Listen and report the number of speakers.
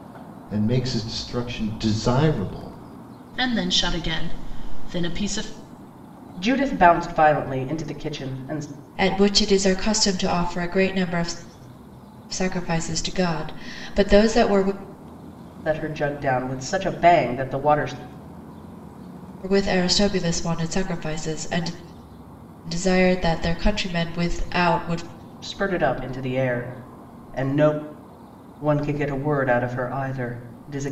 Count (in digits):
4